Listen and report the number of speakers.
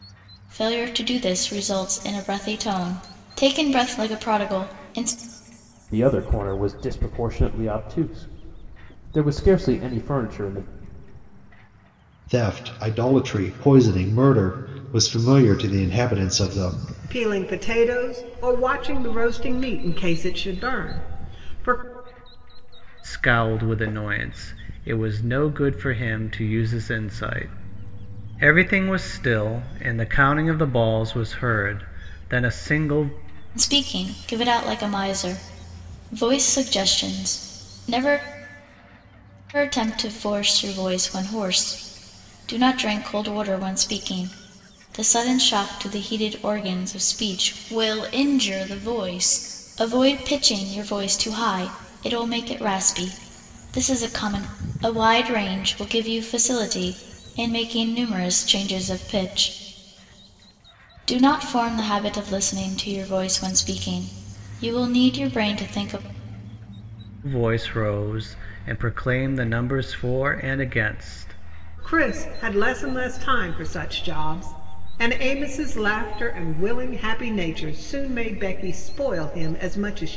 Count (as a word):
five